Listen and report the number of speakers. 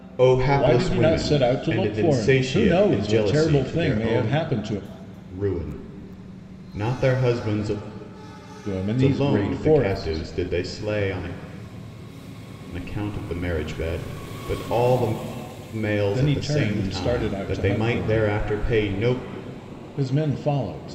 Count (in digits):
2